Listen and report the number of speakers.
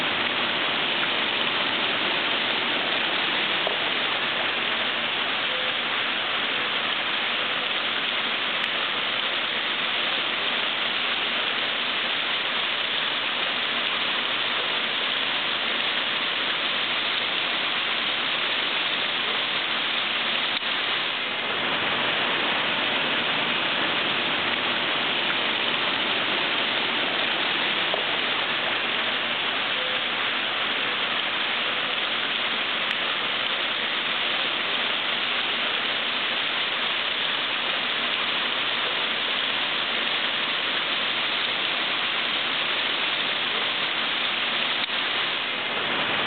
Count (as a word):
zero